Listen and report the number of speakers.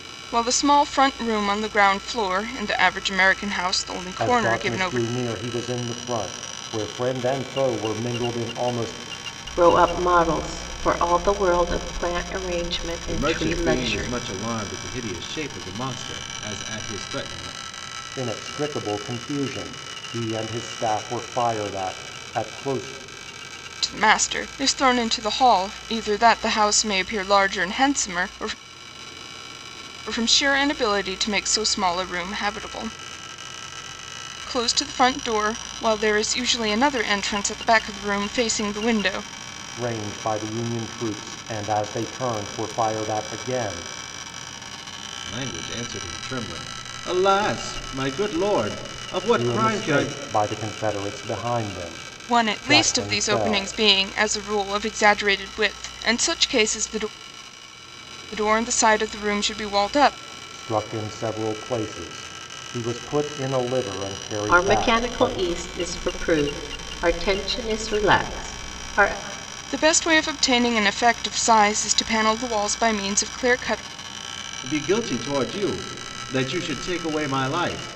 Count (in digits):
4